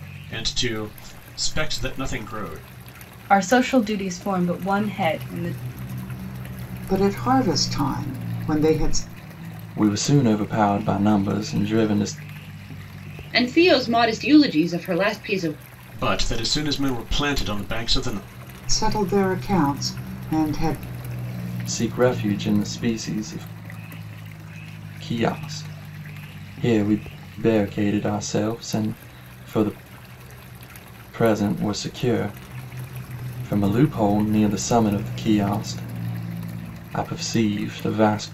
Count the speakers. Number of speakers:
five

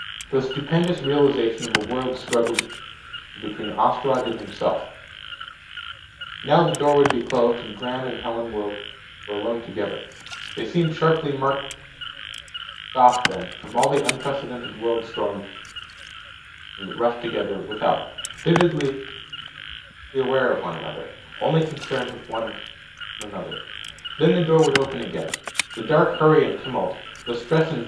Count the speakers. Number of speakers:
one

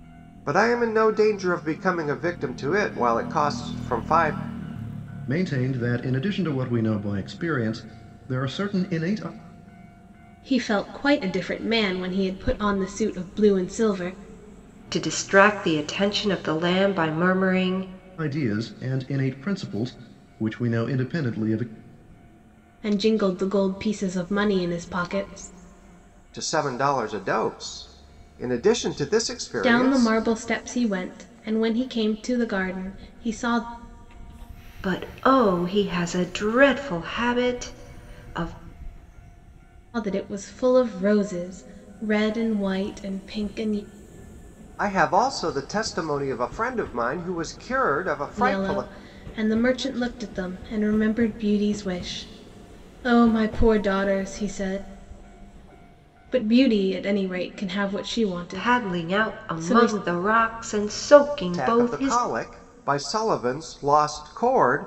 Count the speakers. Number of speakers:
four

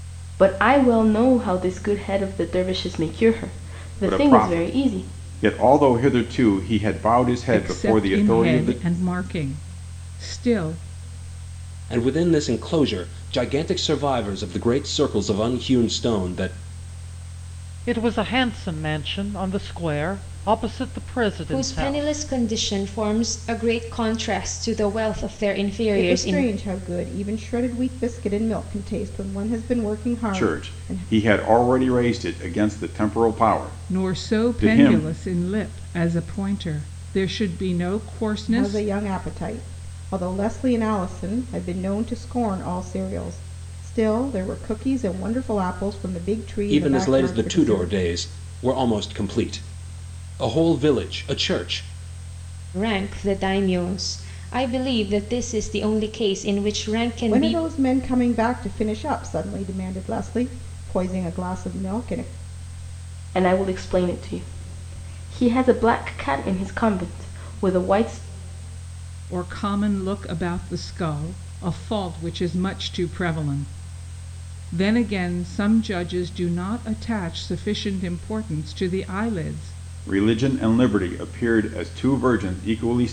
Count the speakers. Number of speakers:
seven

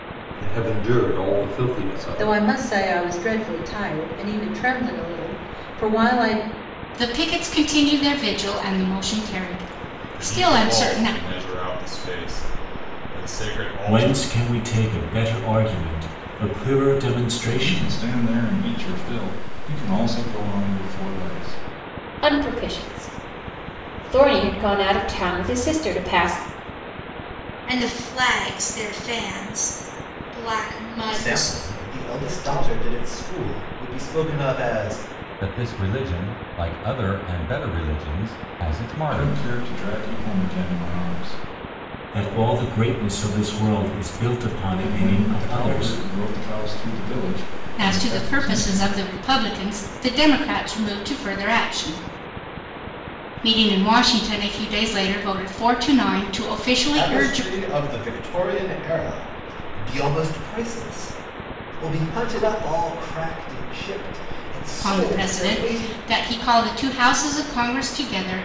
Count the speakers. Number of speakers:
ten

